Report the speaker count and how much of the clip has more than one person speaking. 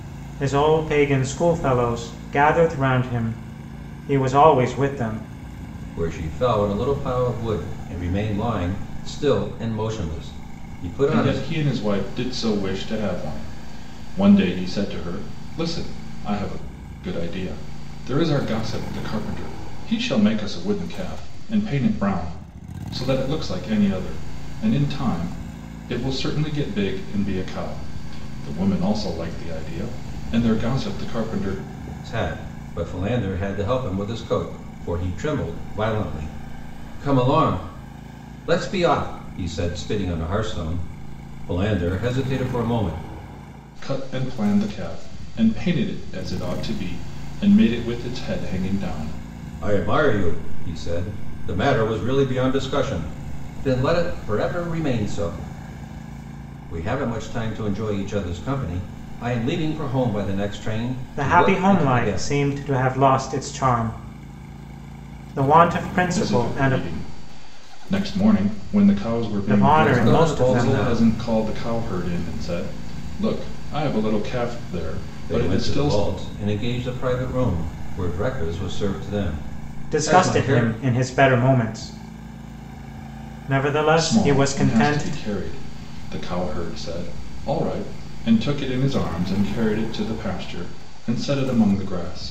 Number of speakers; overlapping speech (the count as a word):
three, about 7%